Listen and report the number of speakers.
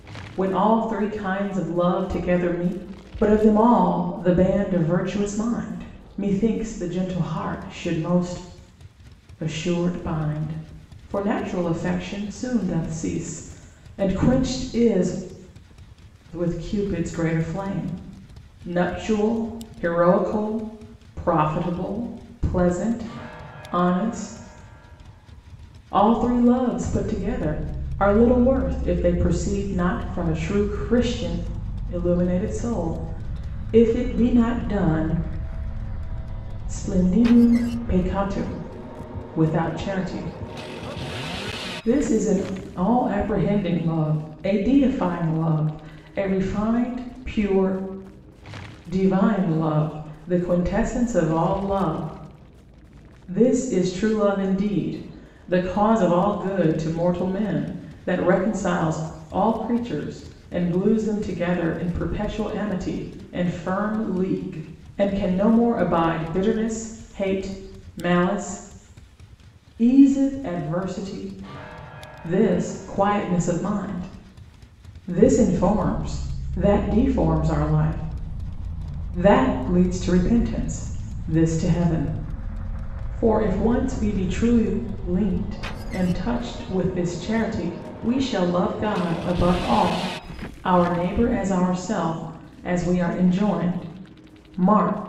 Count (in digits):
1